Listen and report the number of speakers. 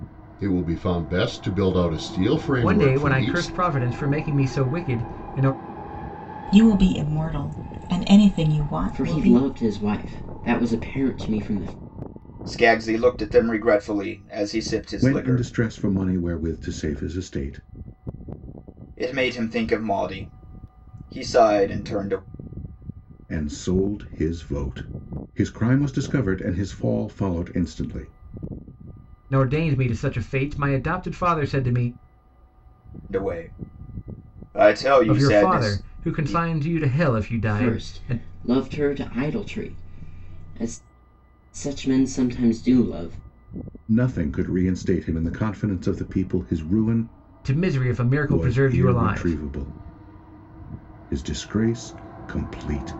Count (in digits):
6